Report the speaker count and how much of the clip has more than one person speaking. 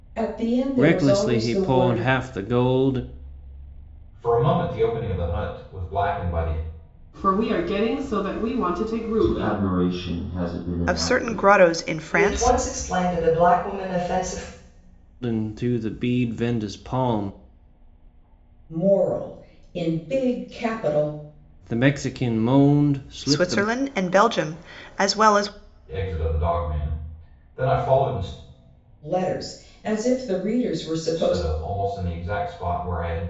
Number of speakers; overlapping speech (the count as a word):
seven, about 11%